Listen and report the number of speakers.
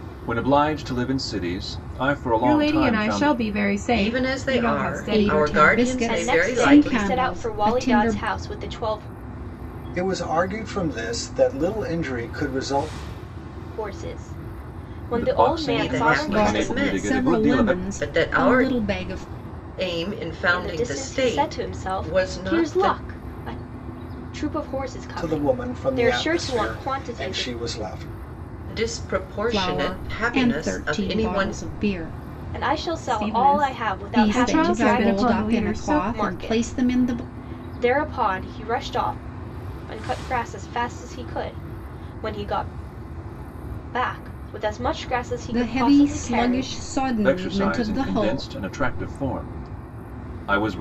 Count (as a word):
six